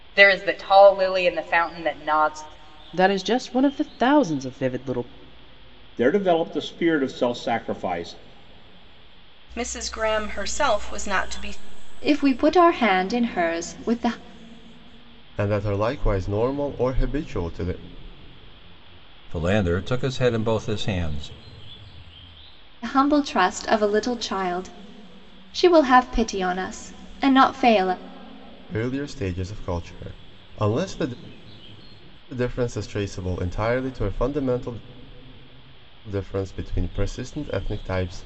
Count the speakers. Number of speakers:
seven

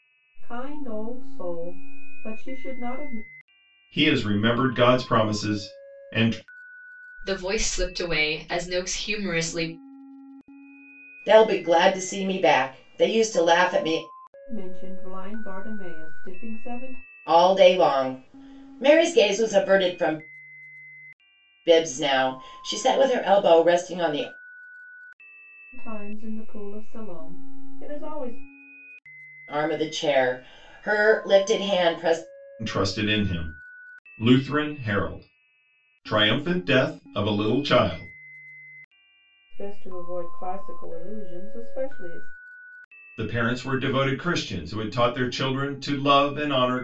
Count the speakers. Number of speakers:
four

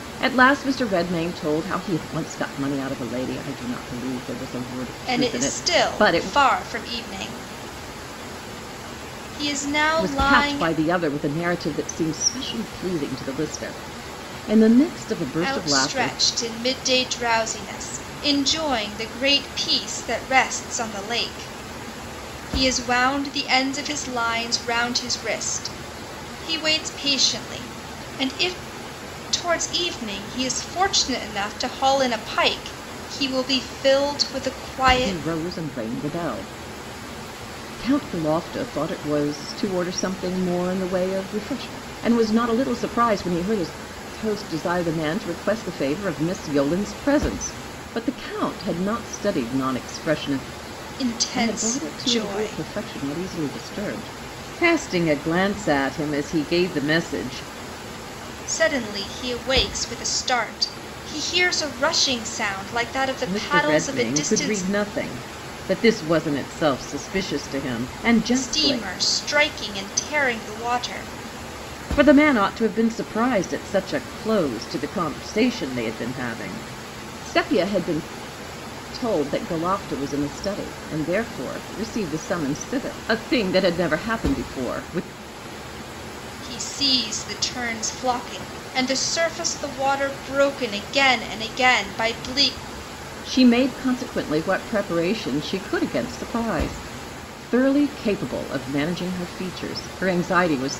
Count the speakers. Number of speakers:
two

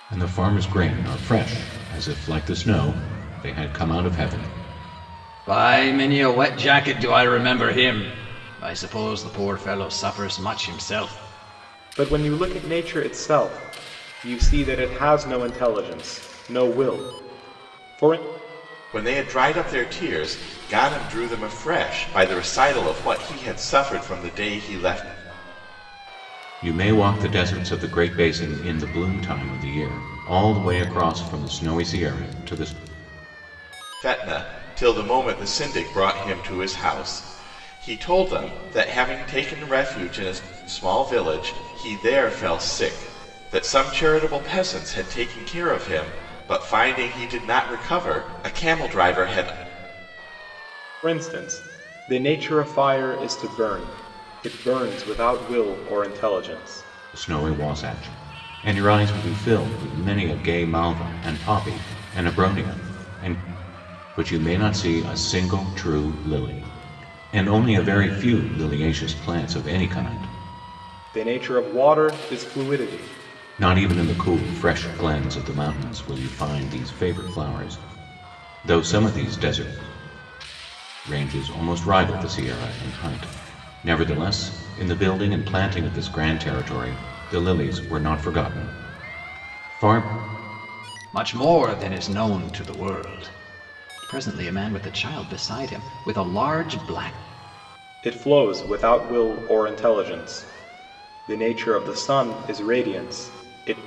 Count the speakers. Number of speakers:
four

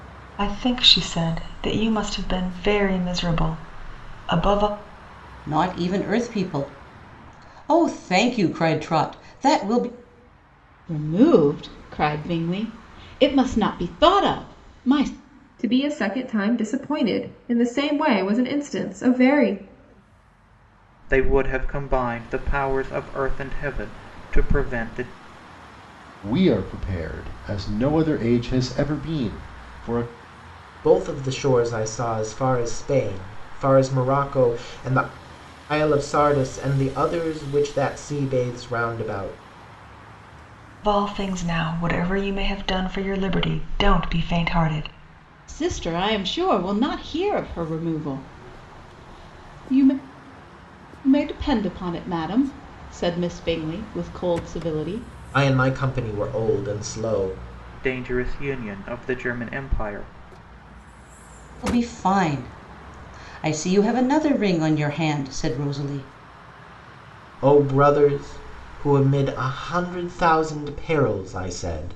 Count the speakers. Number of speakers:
seven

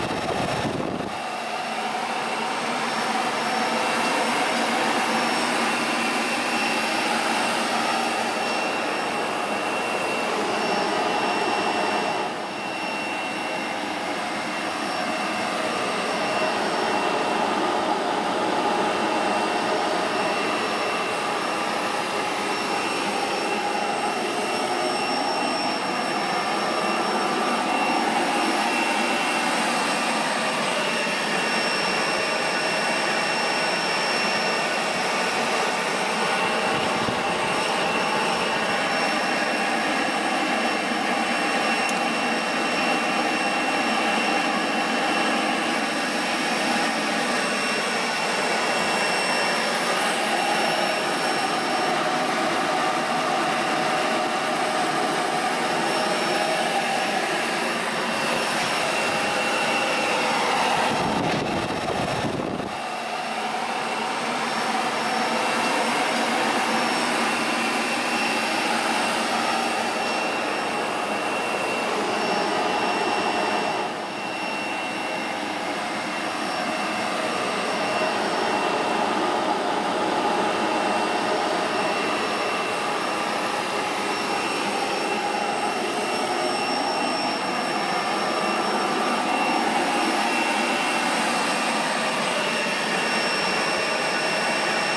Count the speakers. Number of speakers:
zero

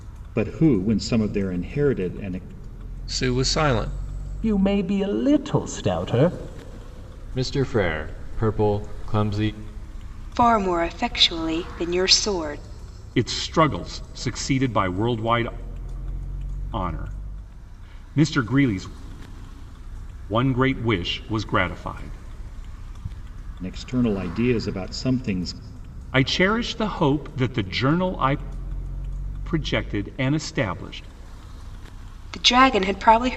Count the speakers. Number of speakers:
six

